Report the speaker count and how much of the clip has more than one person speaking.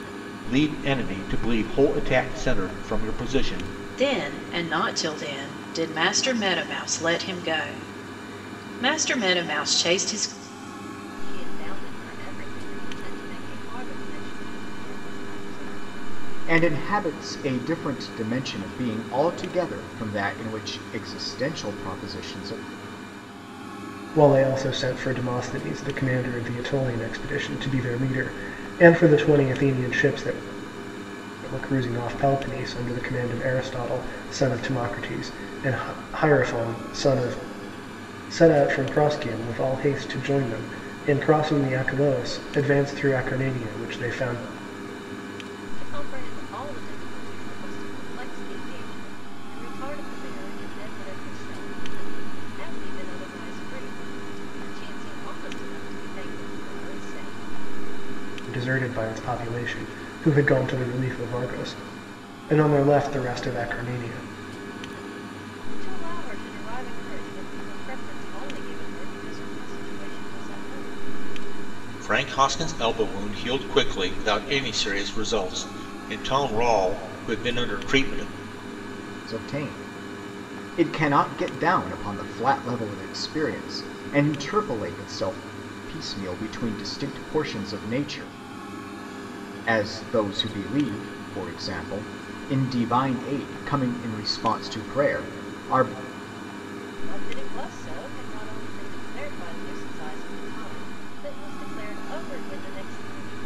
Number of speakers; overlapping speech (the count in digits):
5, no overlap